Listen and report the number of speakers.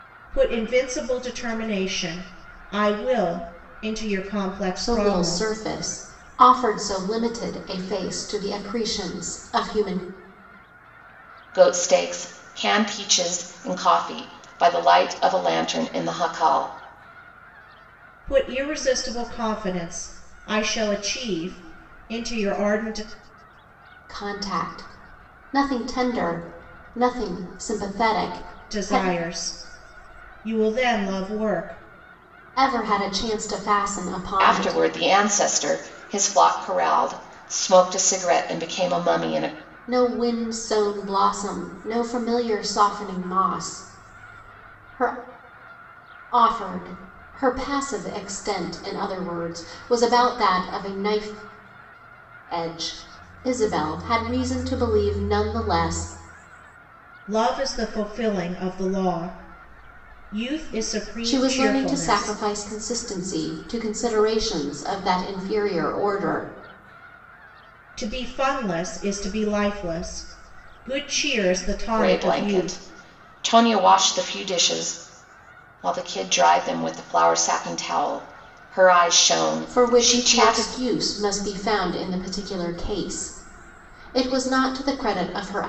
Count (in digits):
3